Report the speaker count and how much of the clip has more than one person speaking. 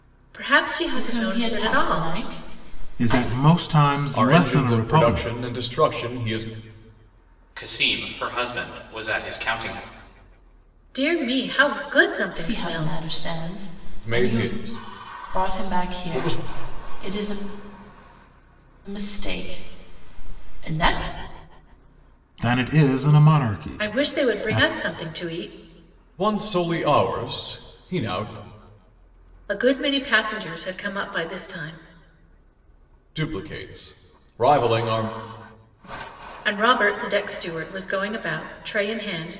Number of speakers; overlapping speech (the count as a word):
five, about 16%